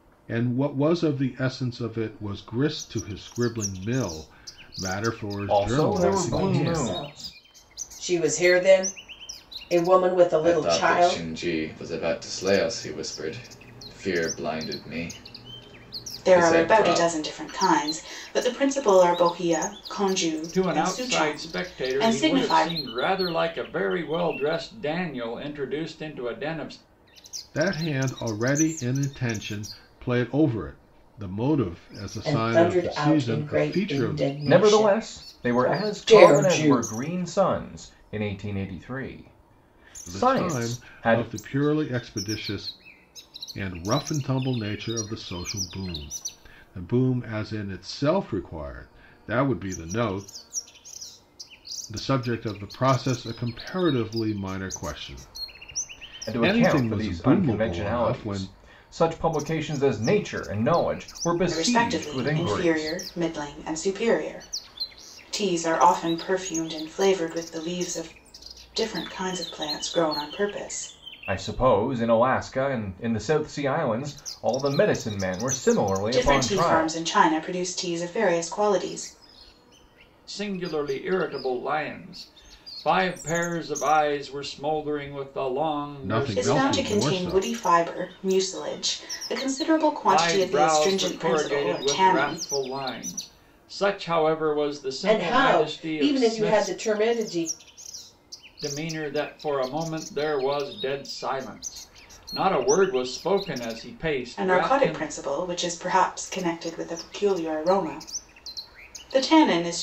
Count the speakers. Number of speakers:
six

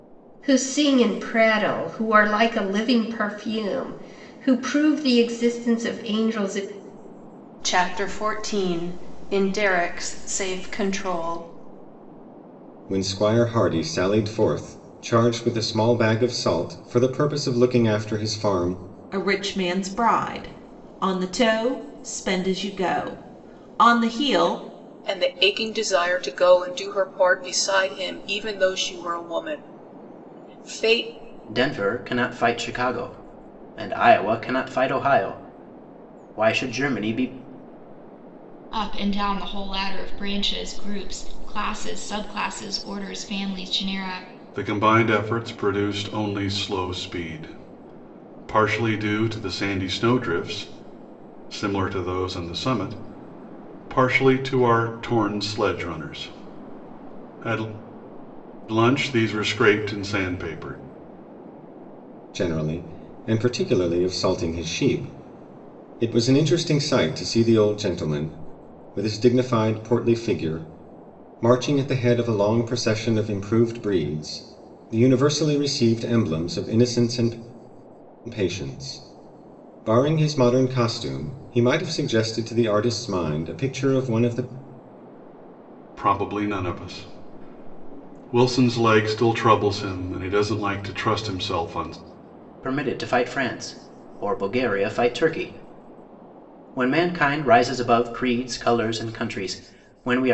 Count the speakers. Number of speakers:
eight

